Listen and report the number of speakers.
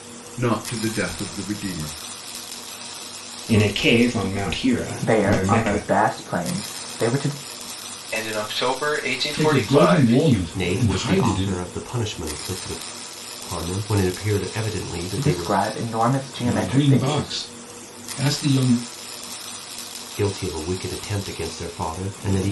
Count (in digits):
6